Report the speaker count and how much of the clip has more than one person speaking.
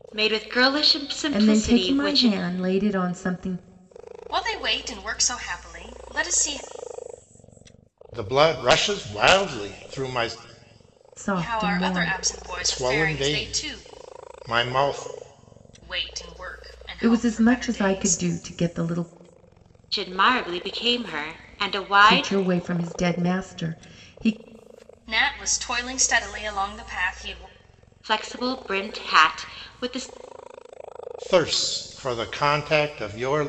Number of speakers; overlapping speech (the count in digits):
4, about 14%